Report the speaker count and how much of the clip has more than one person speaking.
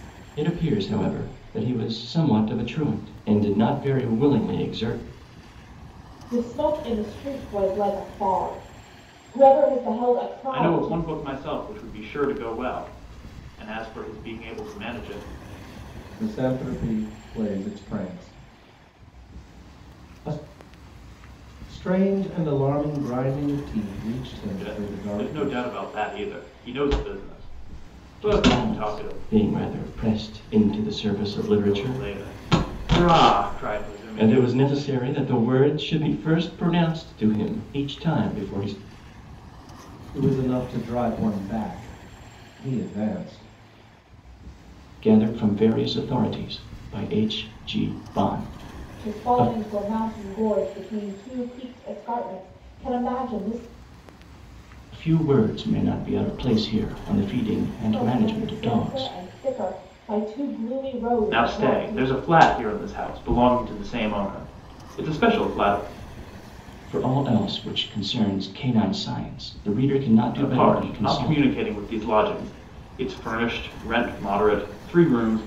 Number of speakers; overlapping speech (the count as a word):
four, about 9%